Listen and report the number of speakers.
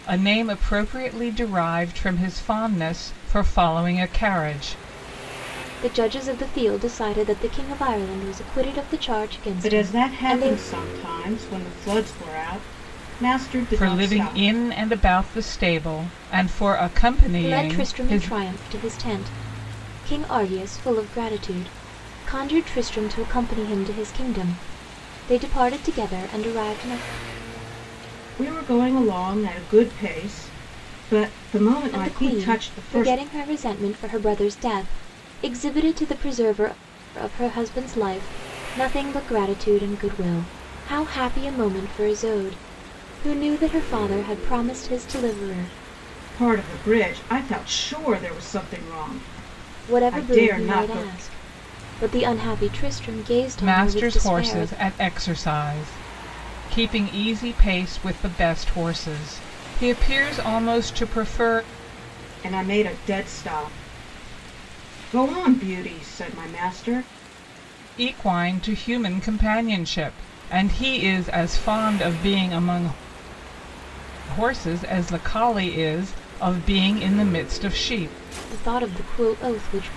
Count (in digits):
3